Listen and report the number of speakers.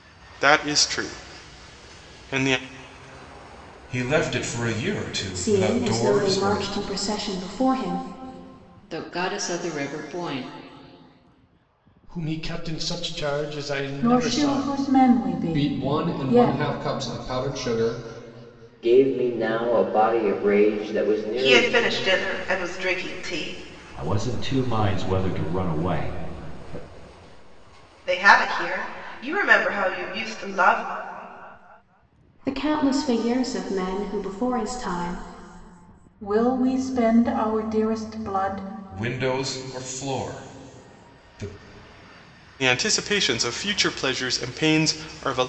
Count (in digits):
10